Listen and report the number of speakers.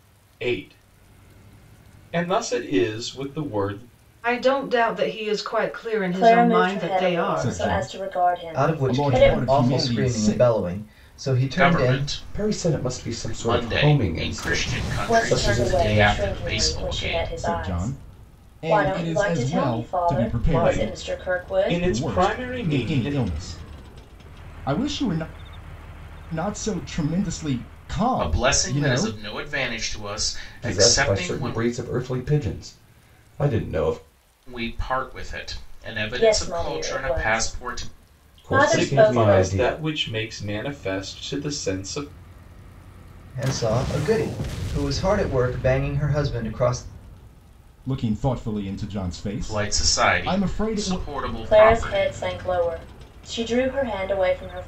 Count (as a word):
seven